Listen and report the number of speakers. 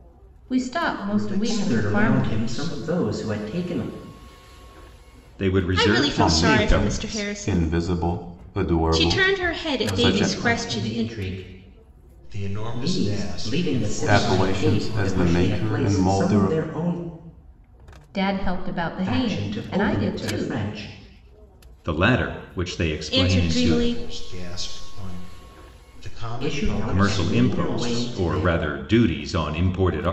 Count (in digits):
6